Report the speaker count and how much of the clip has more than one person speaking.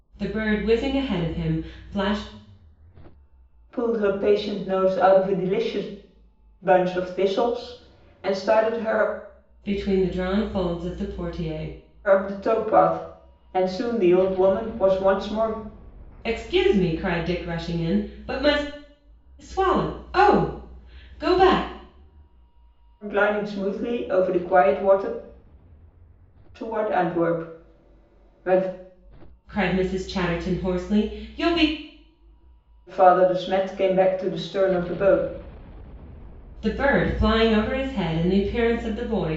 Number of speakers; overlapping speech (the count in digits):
2, no overlap